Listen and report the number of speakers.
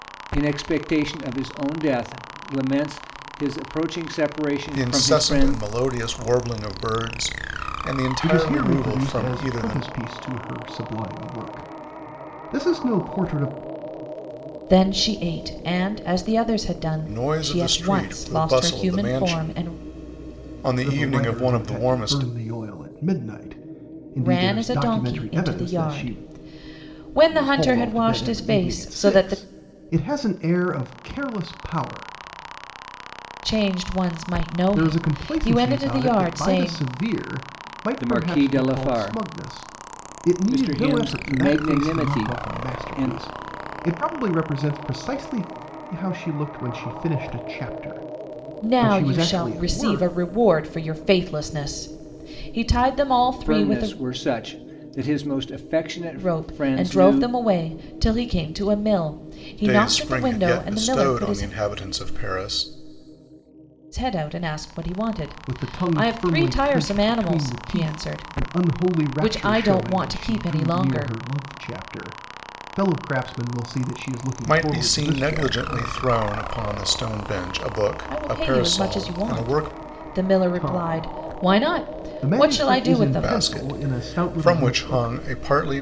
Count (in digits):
4